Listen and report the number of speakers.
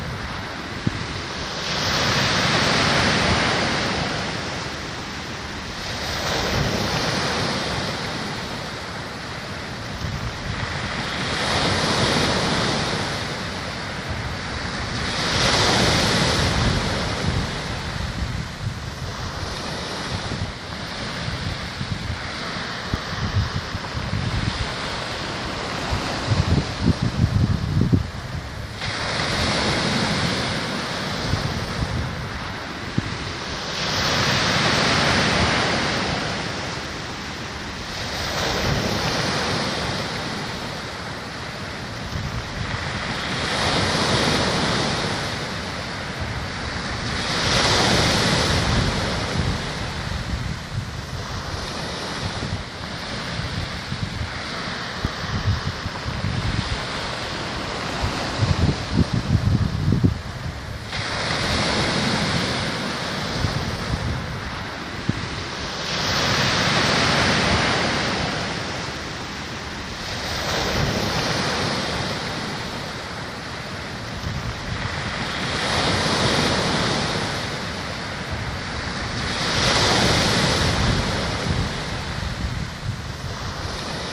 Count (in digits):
0